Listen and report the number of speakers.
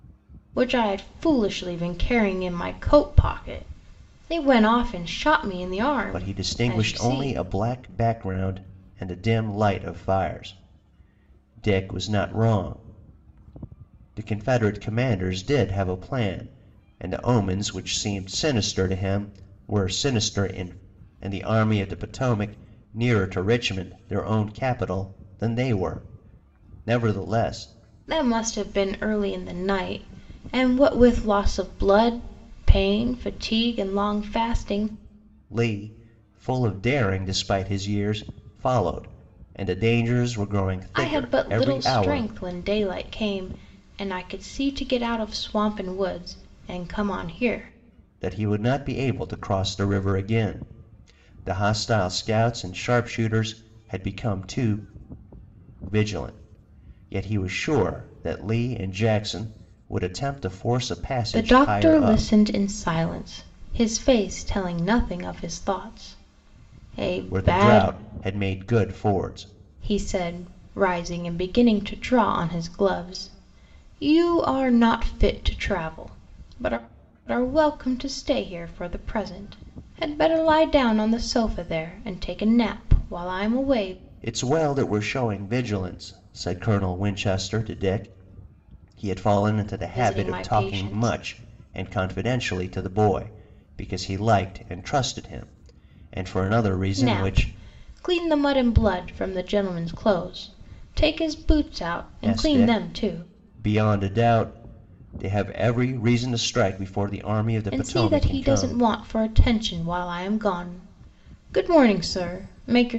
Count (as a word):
two